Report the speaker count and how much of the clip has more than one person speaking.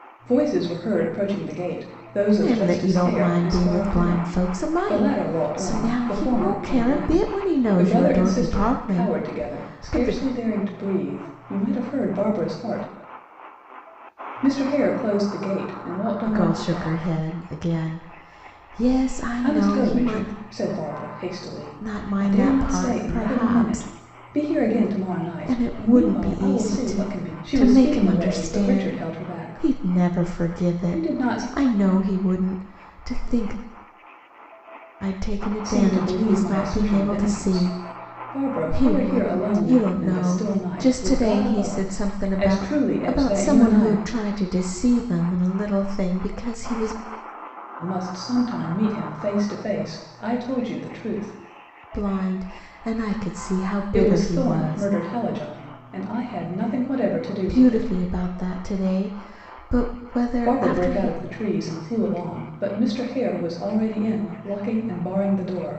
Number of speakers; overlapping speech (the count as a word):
two, about 39%